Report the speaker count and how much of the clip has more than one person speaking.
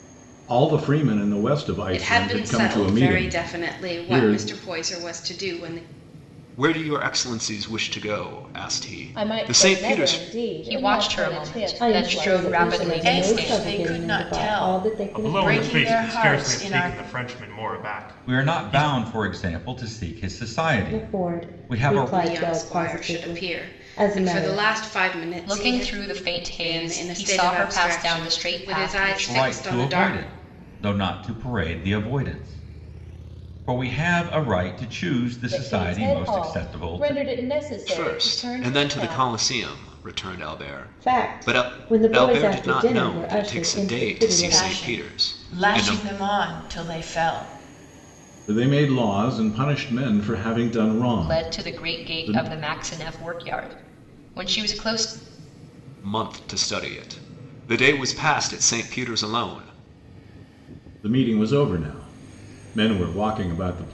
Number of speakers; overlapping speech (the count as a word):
nine, about 43%